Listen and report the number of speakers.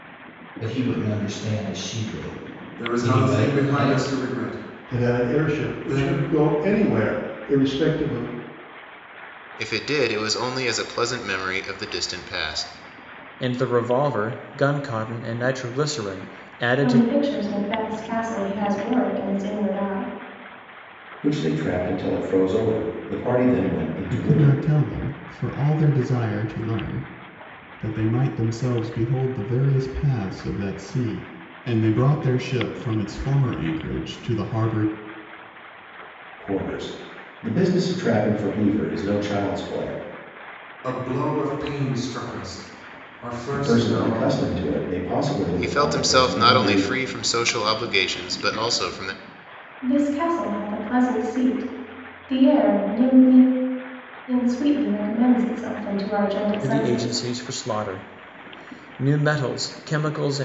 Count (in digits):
8